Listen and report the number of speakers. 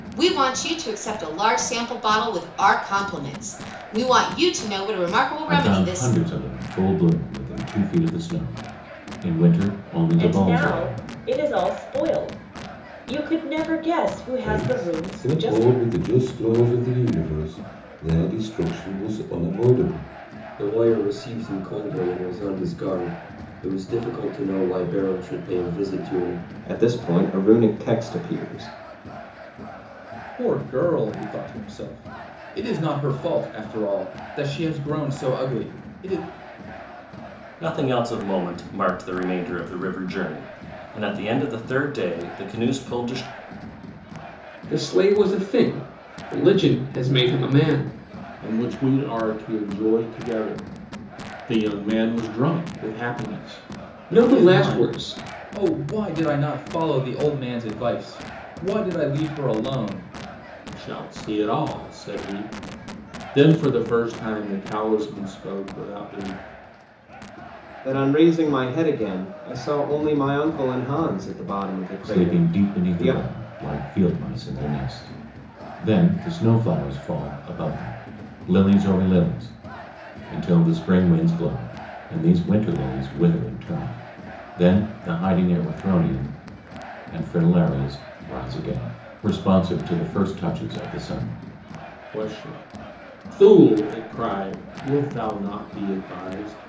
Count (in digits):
10